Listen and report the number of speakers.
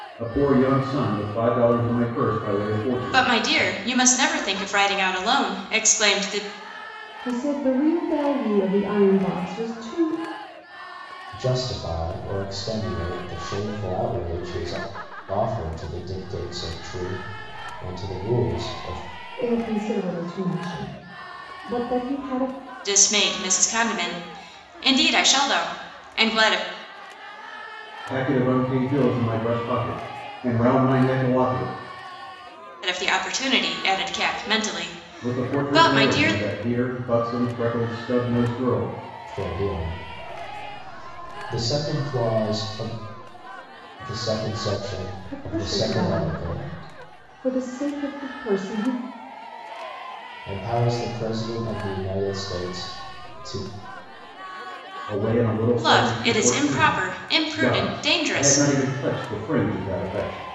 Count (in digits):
4